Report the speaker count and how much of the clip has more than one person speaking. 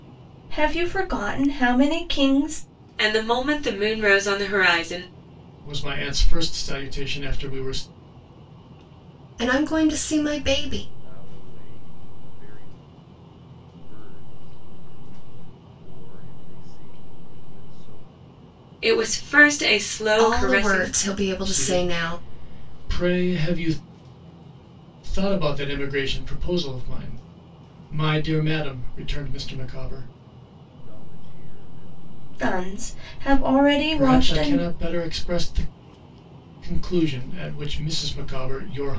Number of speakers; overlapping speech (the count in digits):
5, about 8%